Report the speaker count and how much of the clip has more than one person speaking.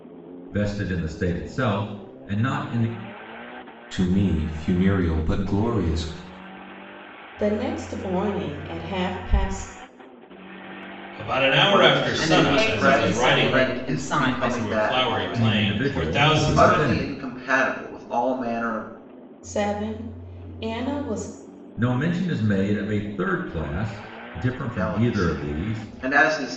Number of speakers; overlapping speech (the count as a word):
six, about 26%